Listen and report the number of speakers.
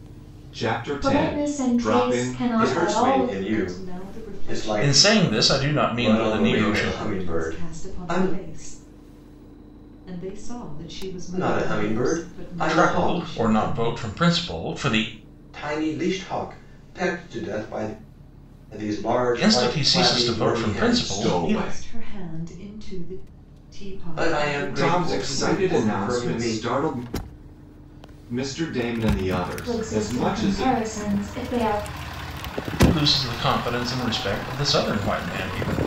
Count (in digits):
5